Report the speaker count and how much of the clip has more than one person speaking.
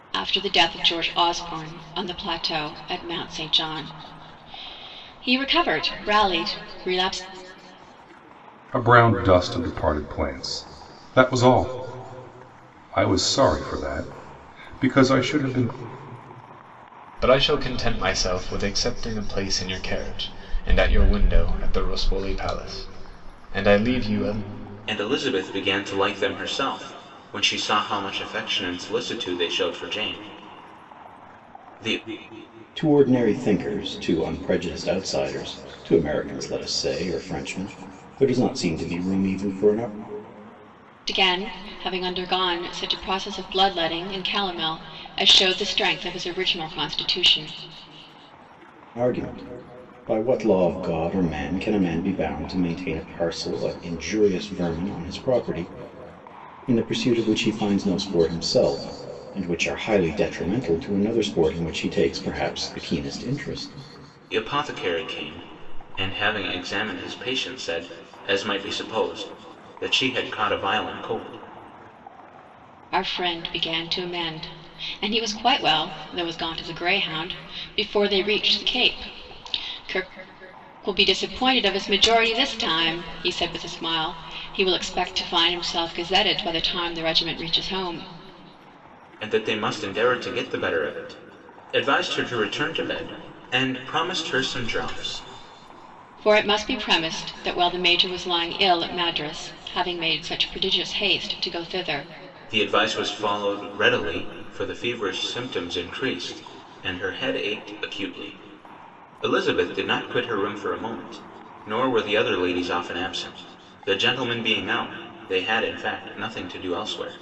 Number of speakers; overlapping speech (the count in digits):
5, no overlap